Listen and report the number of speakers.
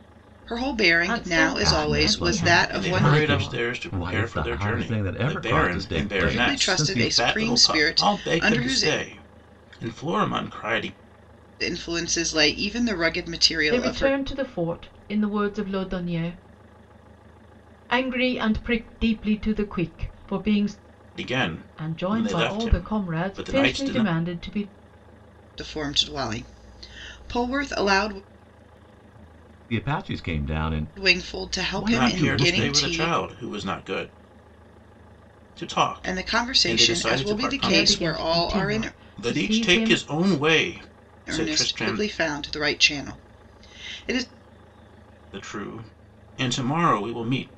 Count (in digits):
4